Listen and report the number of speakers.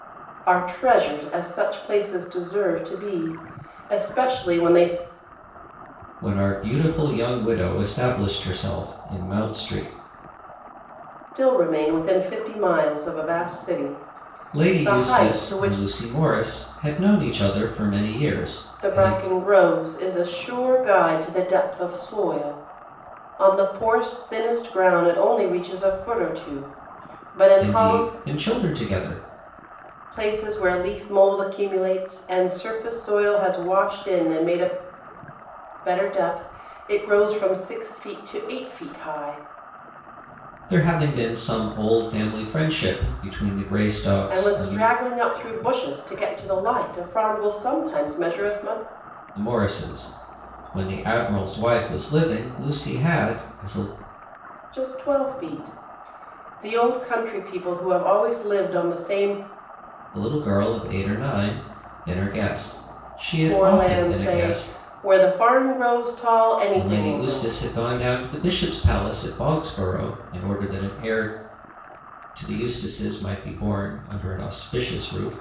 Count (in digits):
2